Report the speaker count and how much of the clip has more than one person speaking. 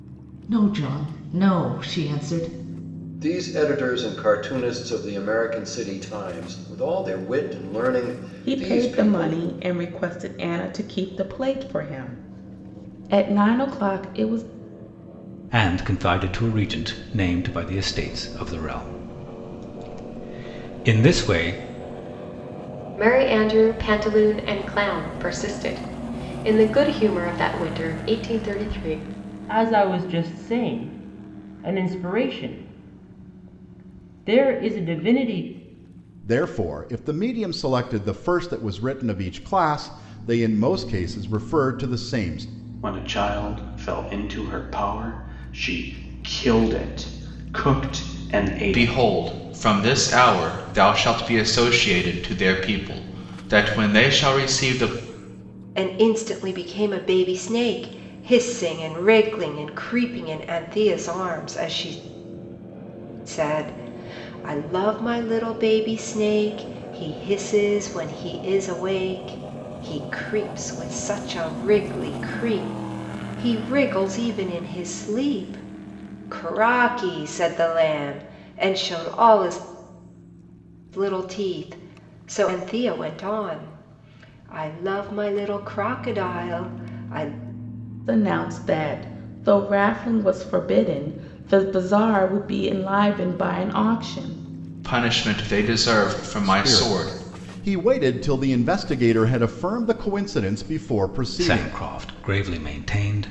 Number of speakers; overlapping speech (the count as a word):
ten, about 2%